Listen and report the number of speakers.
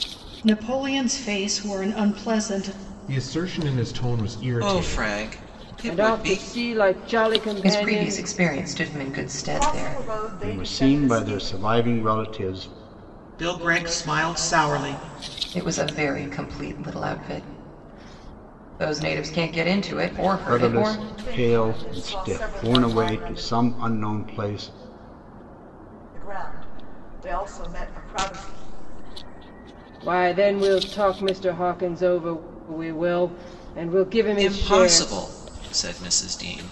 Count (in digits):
8